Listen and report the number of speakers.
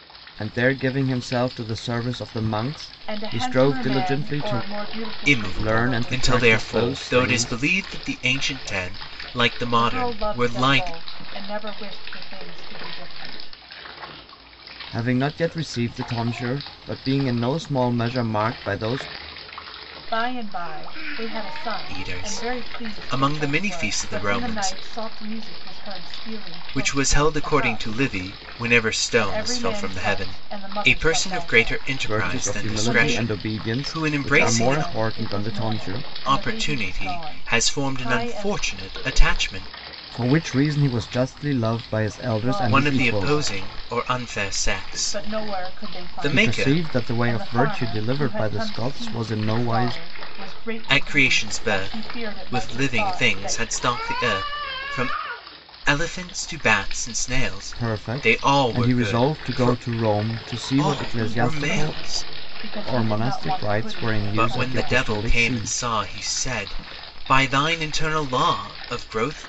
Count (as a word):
three